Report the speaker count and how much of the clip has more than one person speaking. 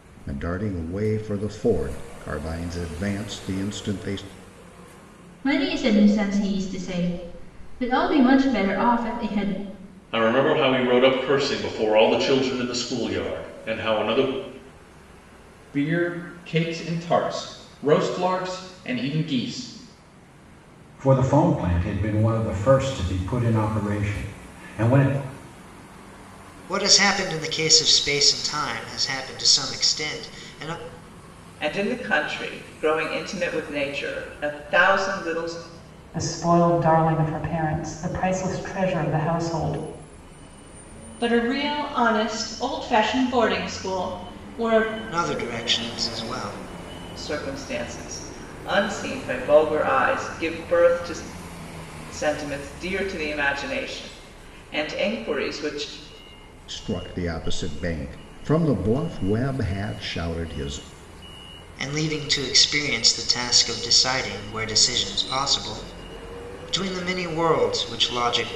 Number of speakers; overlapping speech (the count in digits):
9, no overlap